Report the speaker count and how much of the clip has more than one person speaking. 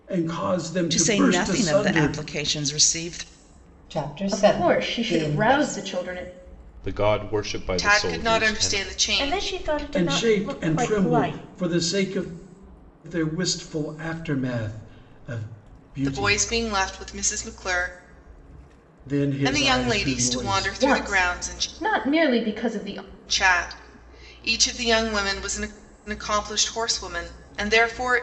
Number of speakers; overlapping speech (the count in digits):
7, about 32%